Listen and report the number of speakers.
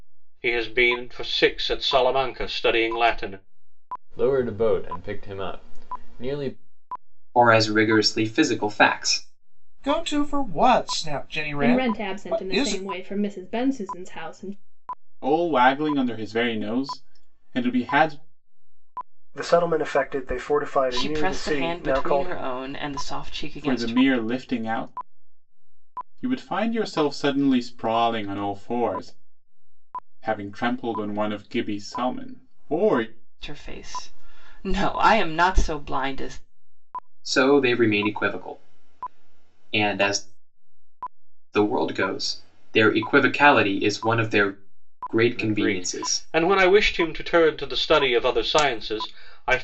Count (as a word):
eight